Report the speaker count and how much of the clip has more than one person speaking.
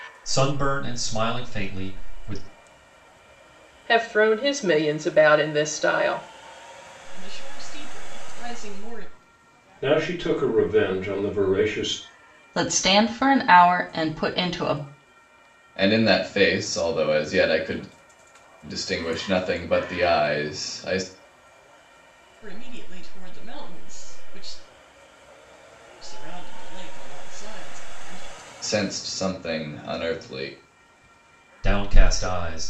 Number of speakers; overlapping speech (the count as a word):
six, no overlap